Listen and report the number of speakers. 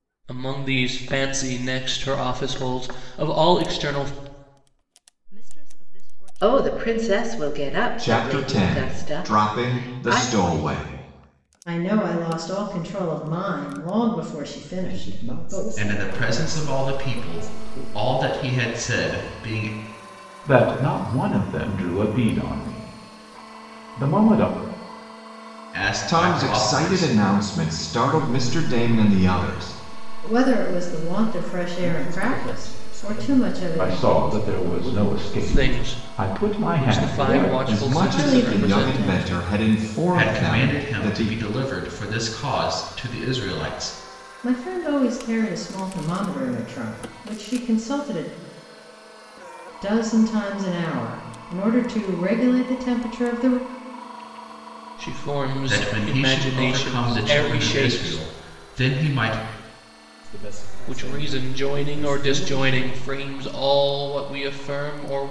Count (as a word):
eight